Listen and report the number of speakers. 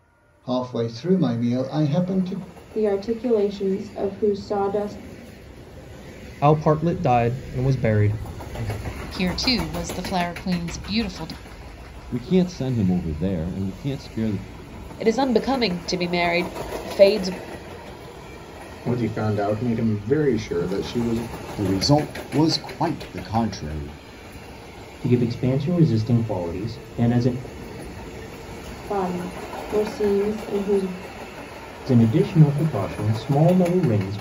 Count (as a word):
nine